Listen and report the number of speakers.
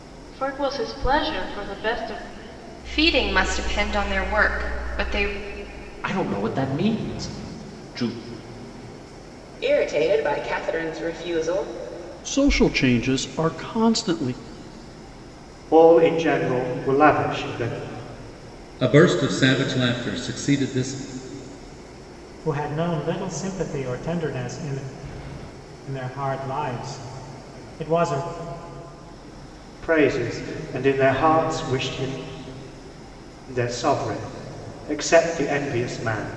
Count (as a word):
eight